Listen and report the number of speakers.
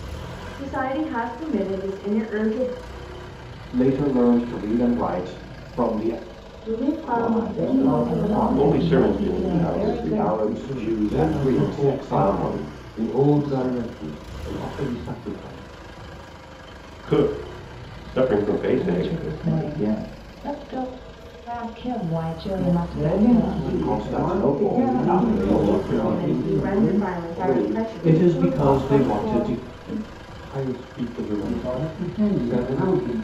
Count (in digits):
8